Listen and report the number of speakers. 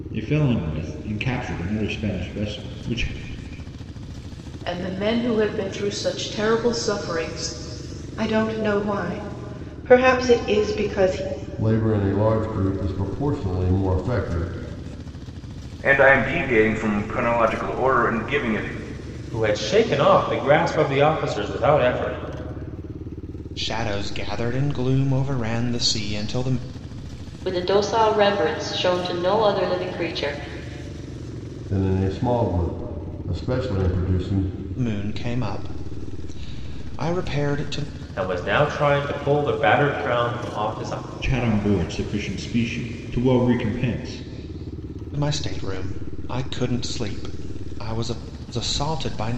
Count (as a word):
eight